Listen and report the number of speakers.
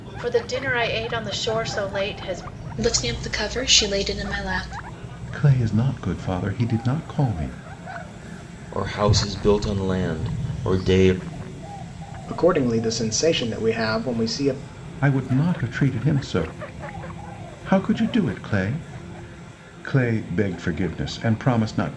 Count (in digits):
5